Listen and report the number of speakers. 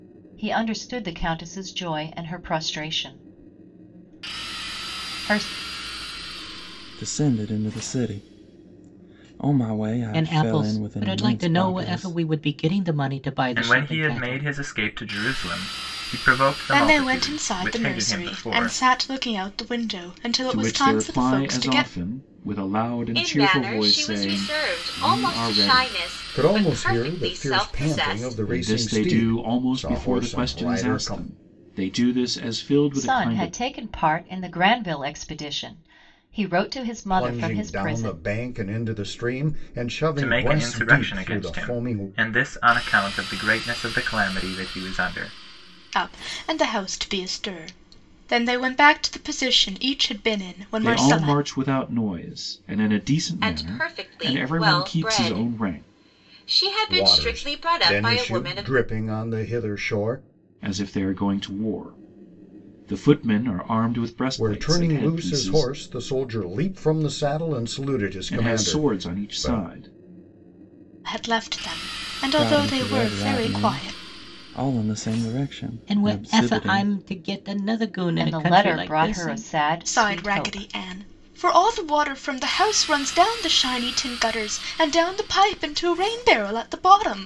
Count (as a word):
eight